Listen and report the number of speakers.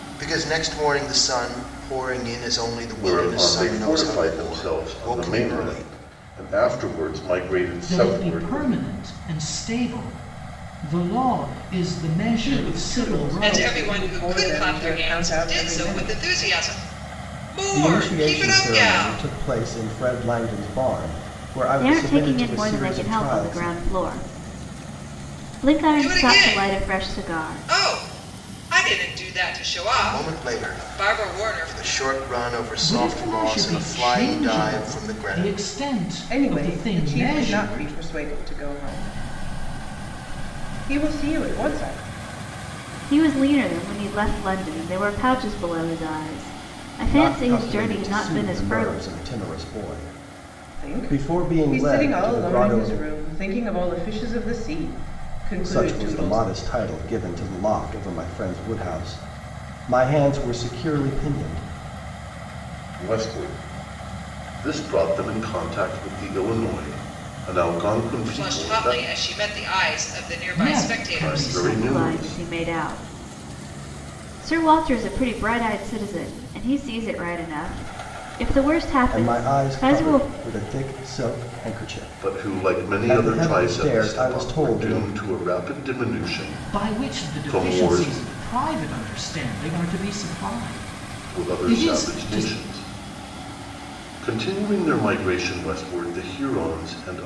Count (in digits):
7